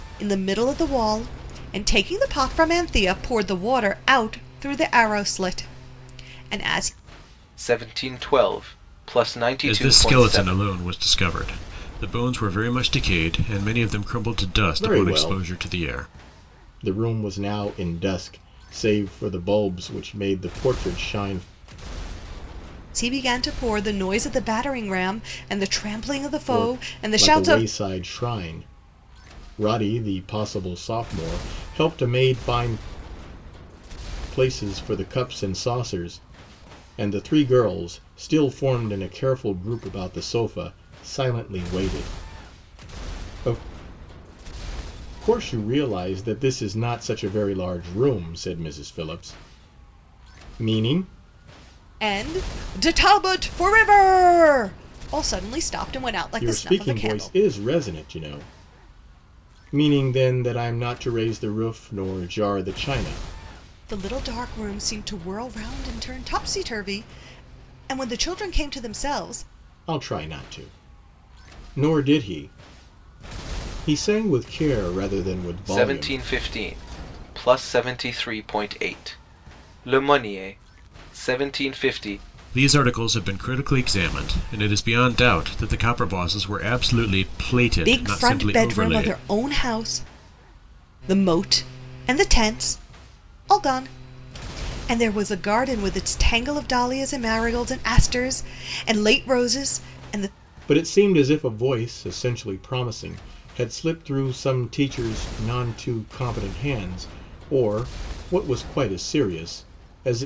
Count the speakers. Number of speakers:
four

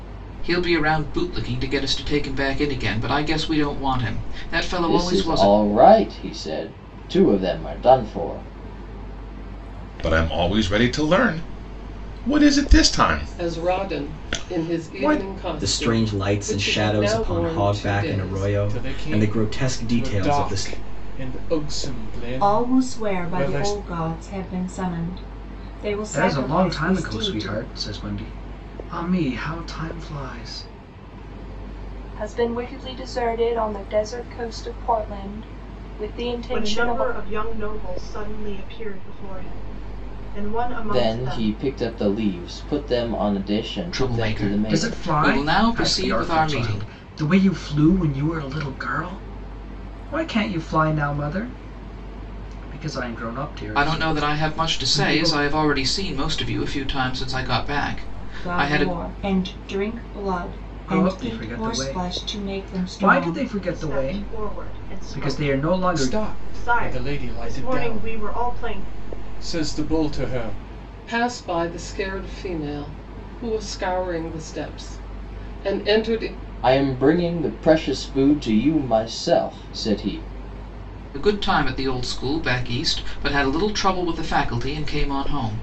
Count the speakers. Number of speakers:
ten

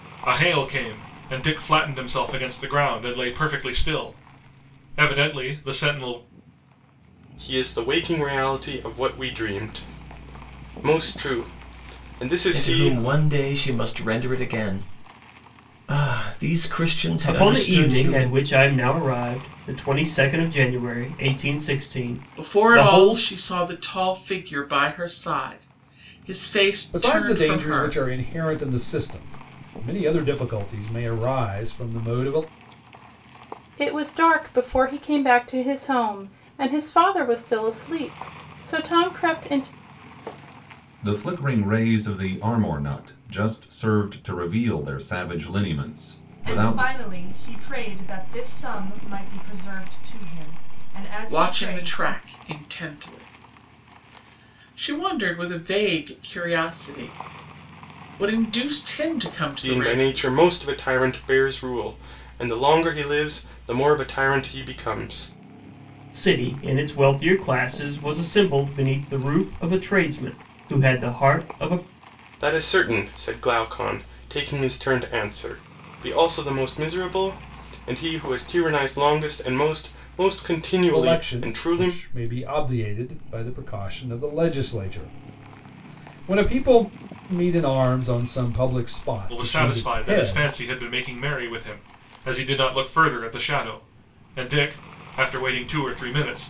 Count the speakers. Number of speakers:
nine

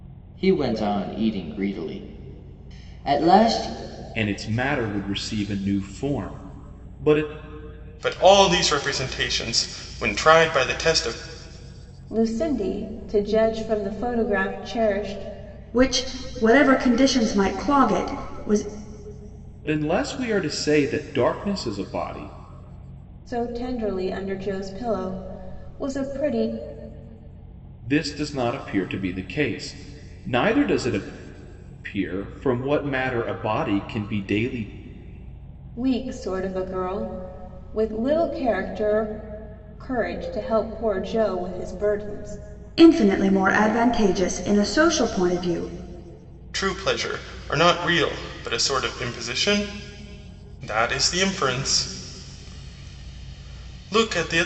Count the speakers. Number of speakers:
five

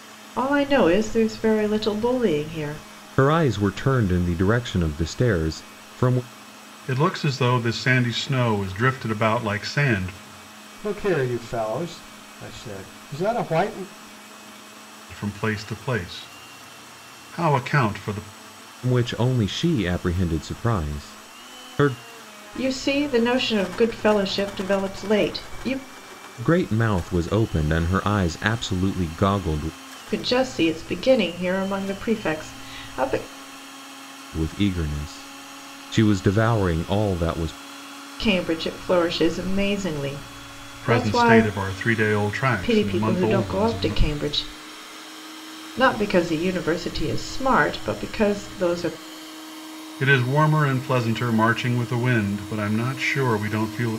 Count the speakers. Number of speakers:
four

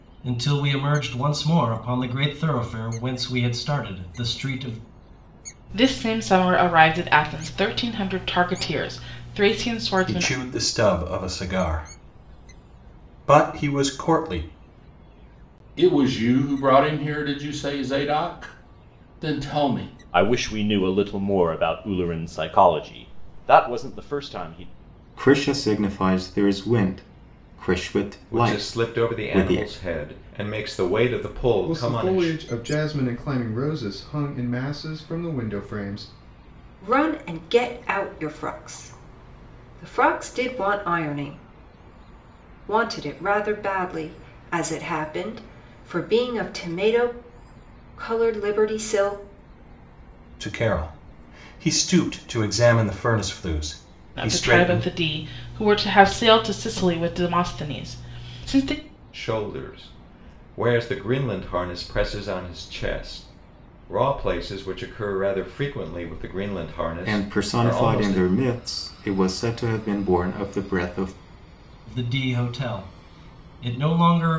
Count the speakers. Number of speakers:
nine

